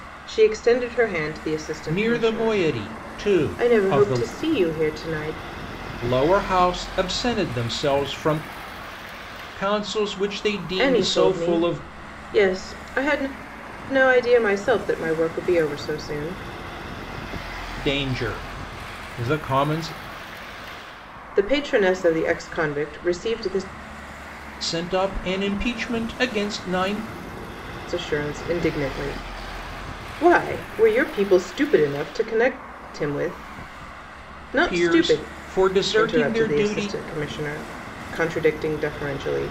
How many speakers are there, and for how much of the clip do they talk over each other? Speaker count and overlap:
2, about 11%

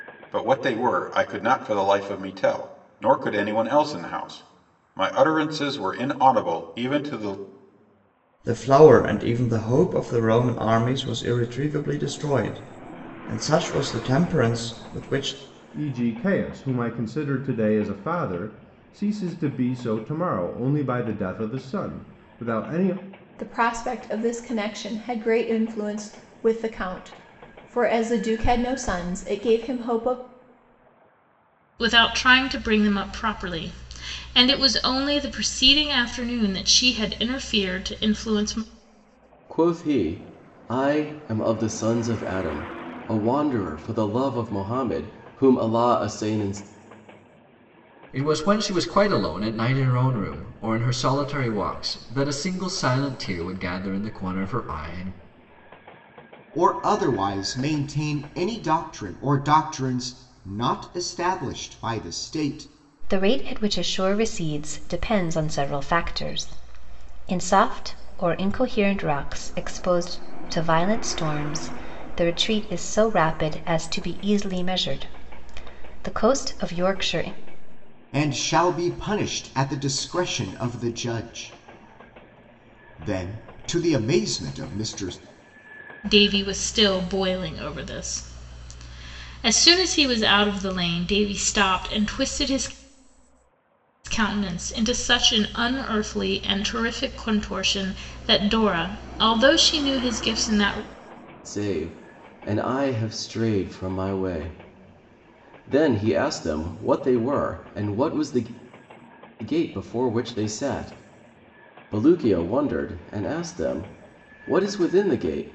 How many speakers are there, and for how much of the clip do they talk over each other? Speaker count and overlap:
9, no overlap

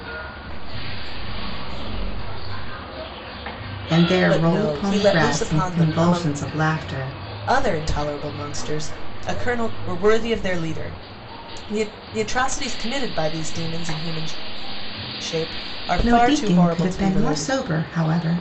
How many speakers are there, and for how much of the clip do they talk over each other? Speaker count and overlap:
3, about 43%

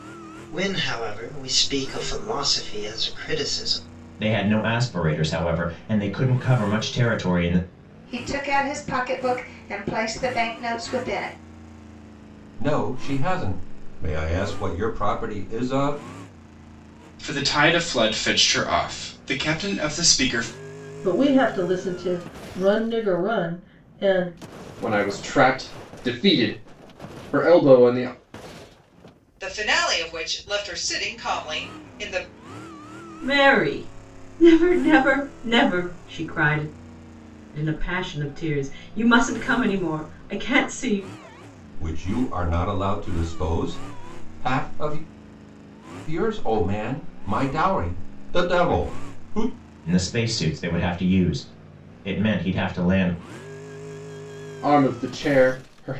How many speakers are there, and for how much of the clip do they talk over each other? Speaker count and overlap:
9, no overlap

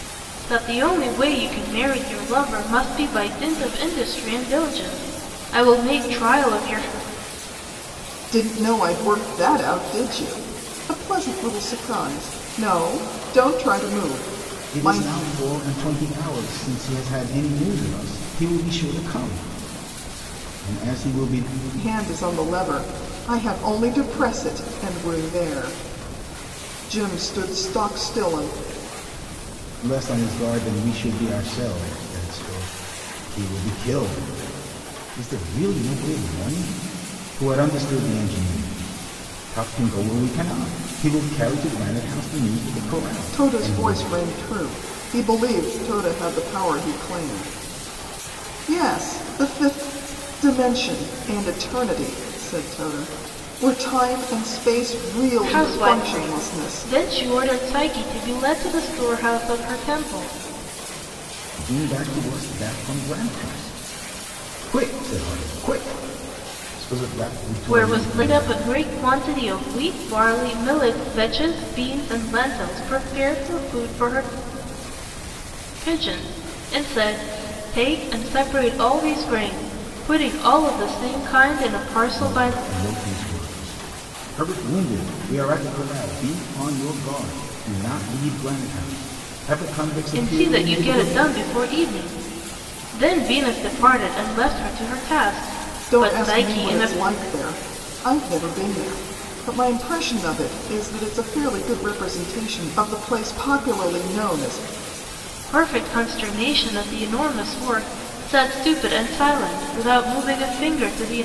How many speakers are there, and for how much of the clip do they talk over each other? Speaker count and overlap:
3, about 6%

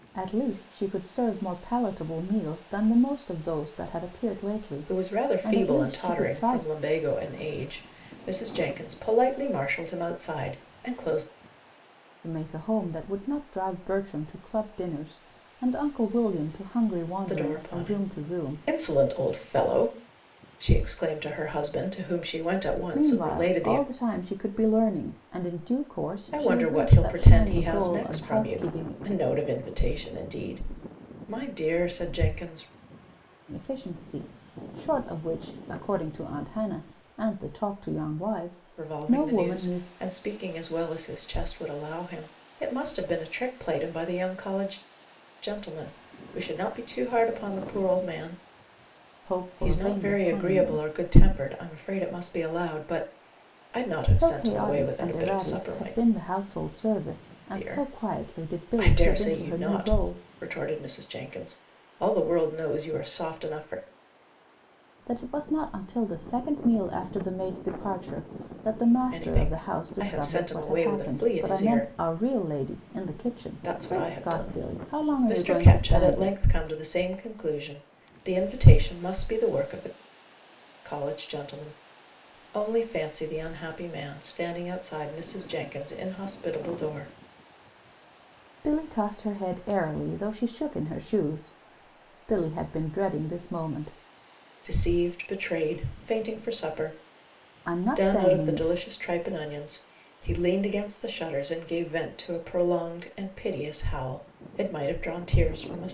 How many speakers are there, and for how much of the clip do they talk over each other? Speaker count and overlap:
2, about 20%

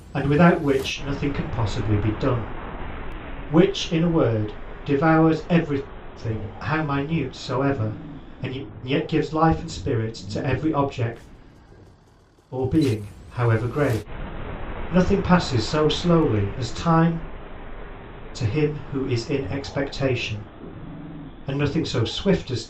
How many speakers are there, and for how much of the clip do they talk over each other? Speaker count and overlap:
1, no overlap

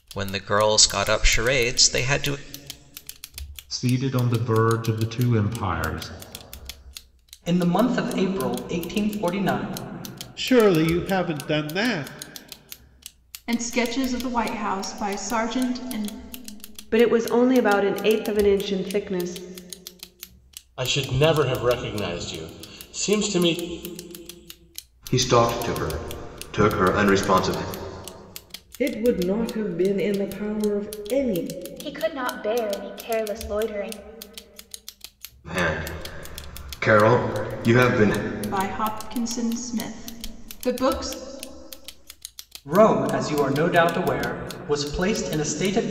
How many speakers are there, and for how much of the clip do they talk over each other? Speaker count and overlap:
10, no overlap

